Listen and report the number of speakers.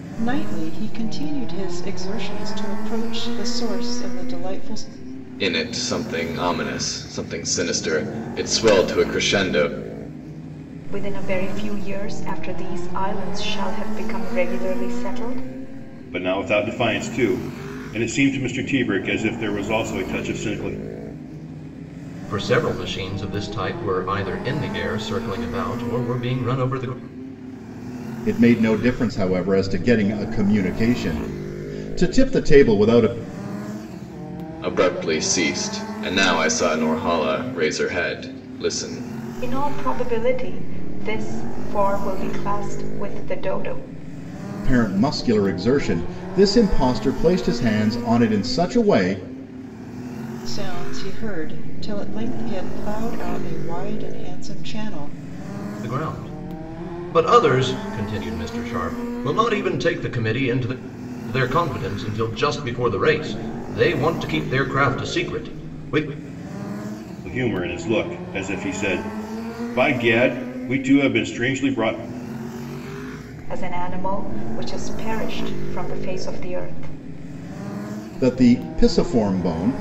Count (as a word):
six